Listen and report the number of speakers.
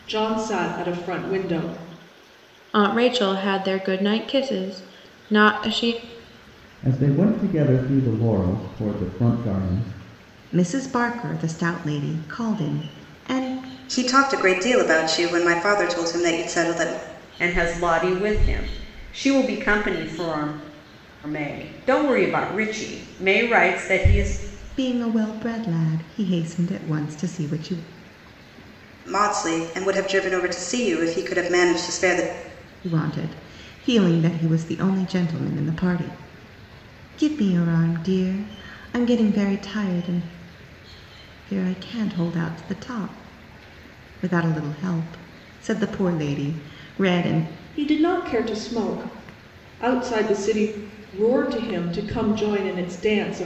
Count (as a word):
six